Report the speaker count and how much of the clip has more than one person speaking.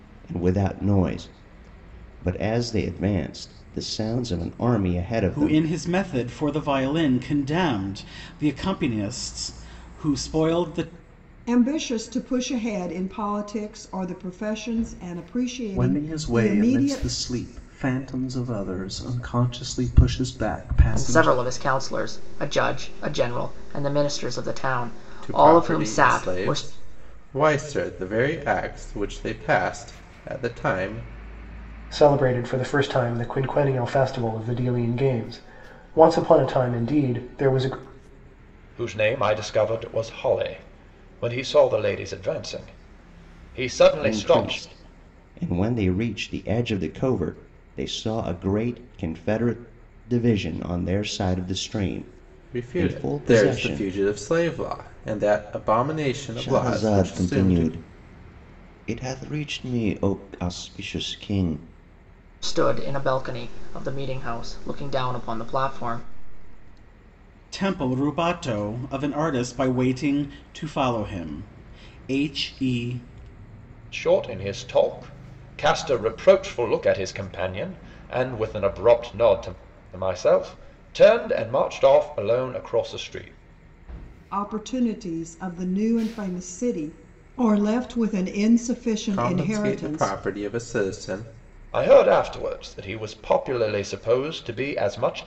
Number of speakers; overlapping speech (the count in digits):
8, about 9%